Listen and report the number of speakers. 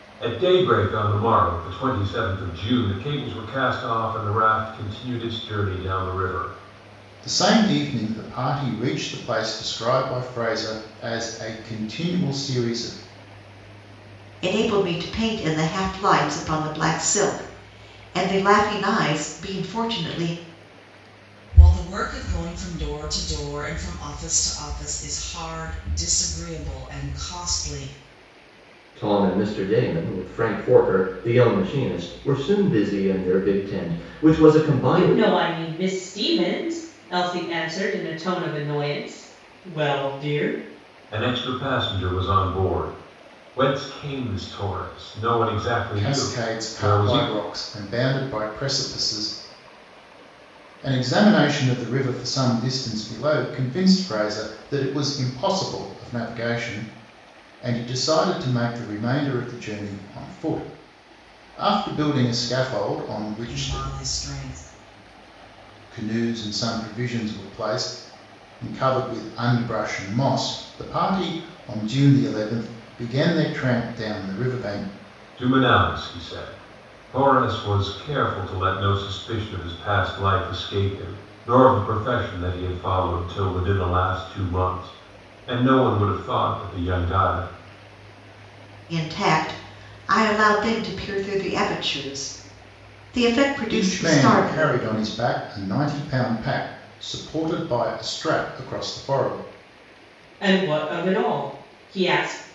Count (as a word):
six